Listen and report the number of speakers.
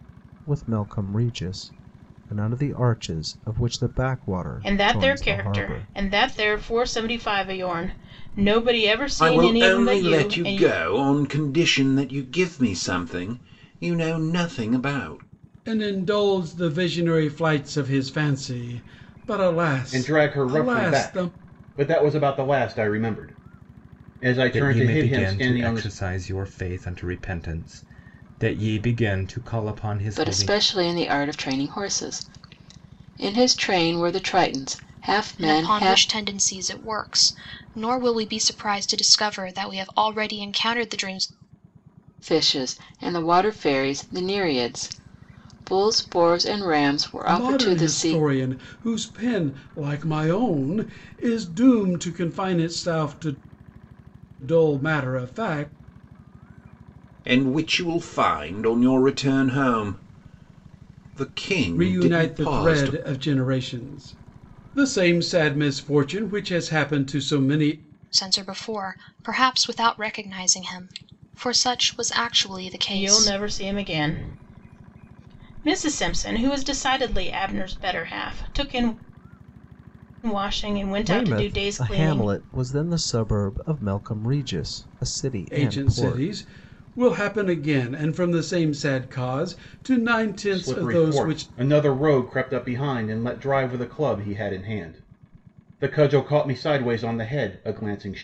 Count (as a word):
eight